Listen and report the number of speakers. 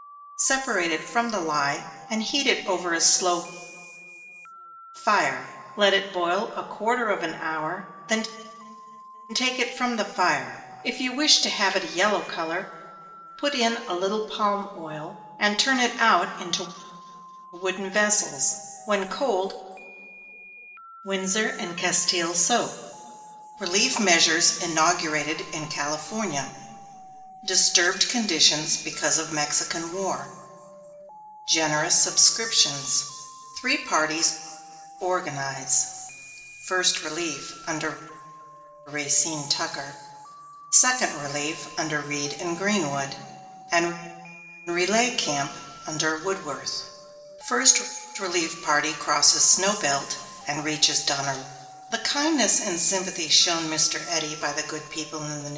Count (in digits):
1